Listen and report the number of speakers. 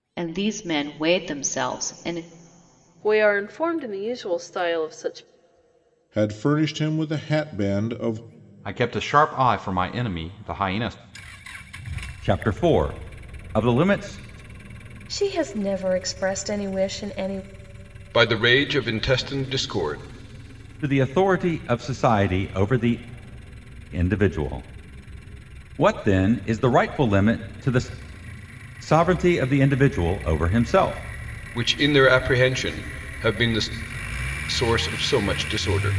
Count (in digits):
7